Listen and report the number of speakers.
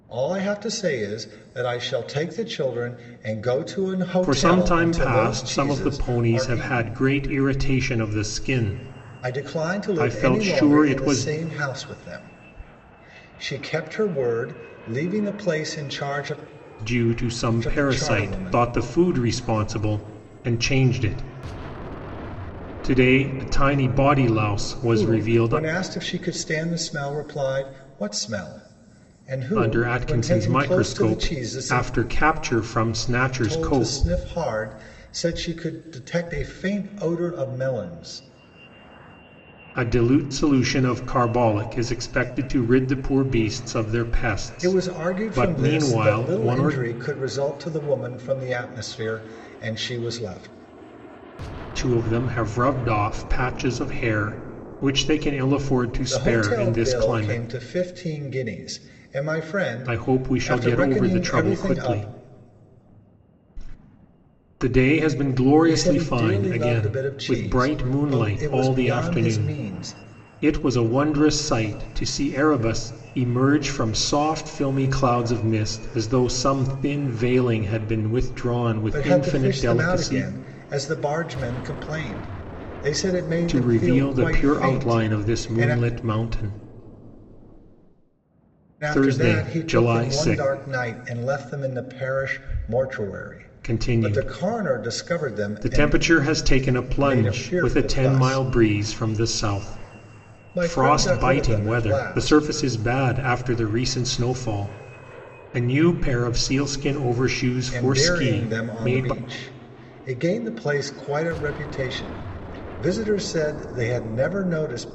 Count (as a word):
two